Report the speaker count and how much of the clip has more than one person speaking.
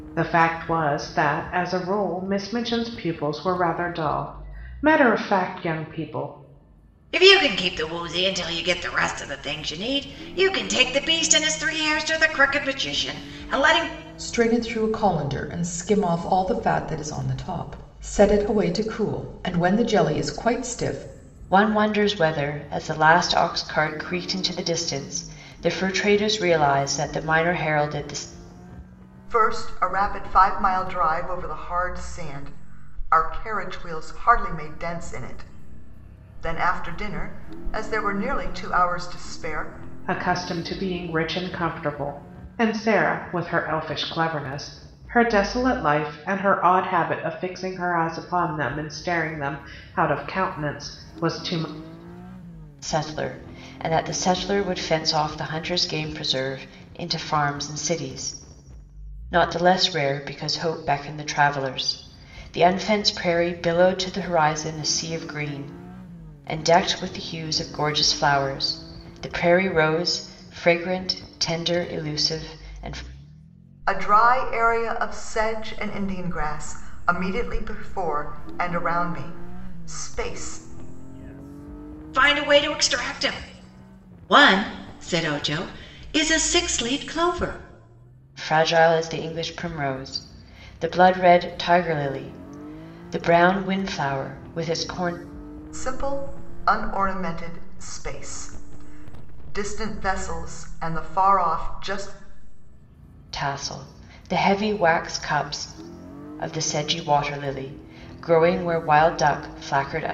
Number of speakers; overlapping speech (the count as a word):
five, no overlap